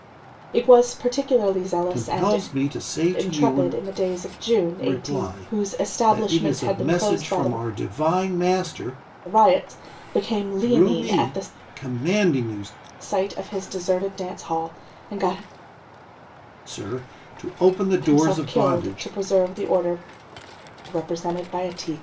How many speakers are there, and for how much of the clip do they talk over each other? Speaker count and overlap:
2, about 27%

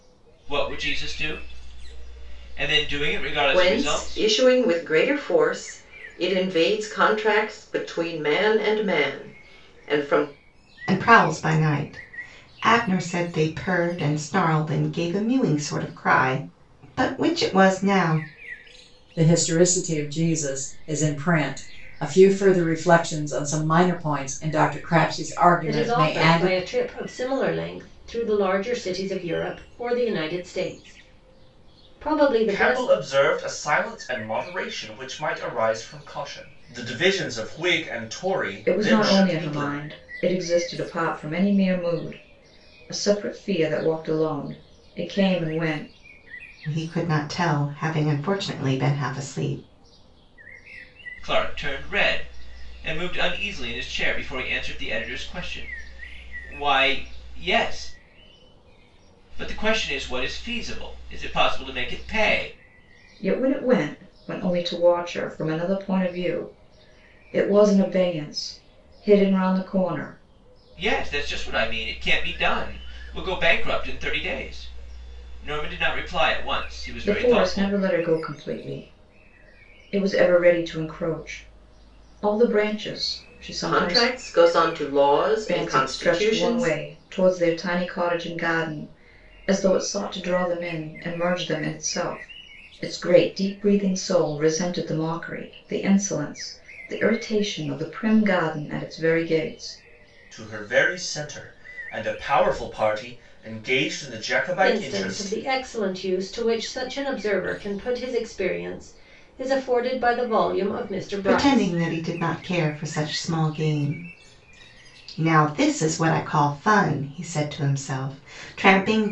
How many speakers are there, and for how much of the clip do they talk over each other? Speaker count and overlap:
7, about 6%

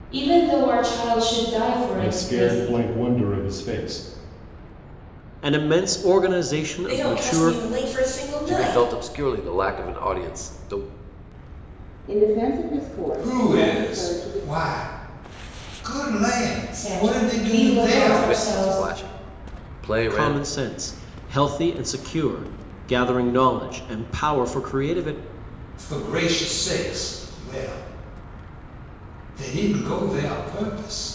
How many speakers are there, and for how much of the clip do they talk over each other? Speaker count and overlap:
7, about 19%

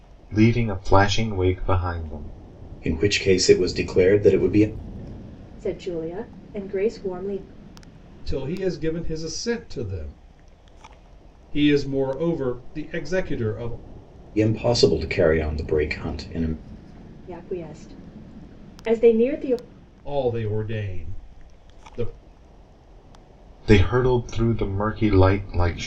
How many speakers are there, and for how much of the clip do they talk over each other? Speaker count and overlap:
4, no overlap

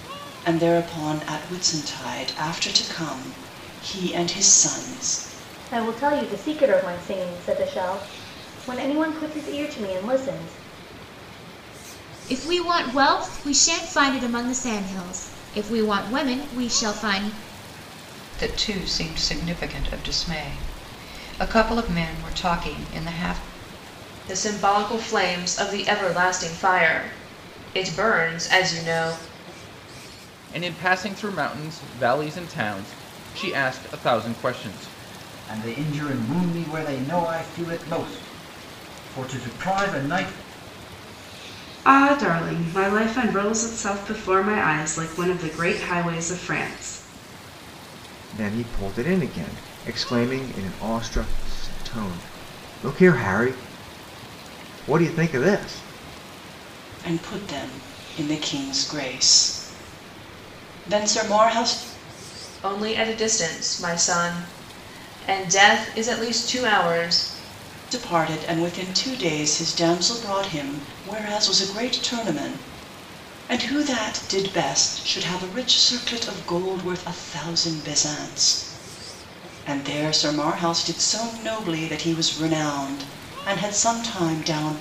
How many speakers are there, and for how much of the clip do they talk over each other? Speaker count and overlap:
9, no overlap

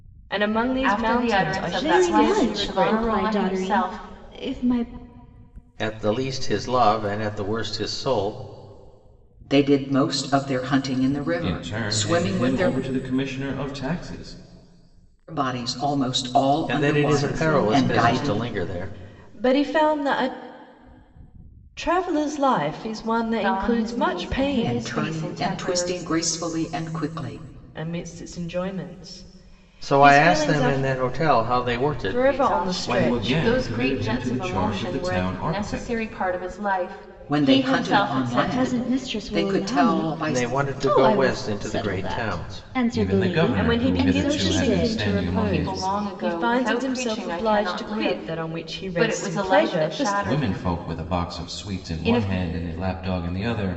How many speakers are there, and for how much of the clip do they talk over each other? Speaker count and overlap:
6, about 53%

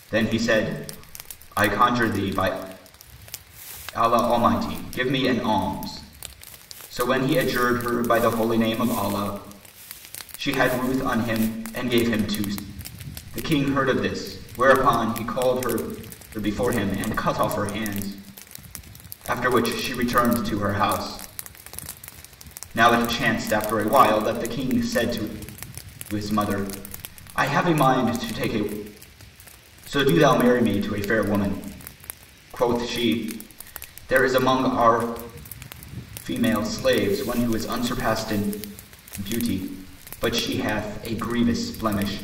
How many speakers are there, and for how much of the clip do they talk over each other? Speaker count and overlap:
1, no overlap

